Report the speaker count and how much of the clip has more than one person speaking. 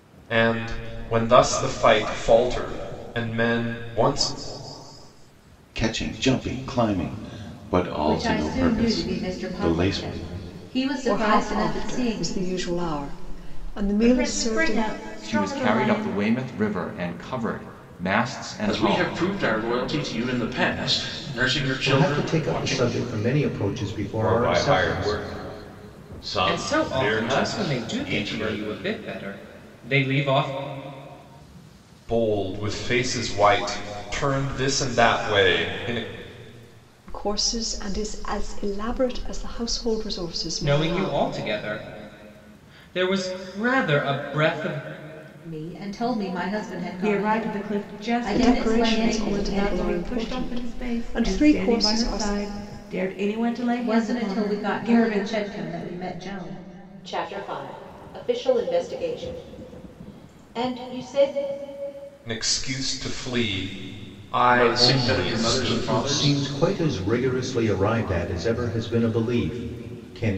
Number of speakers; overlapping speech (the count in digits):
10, about 28%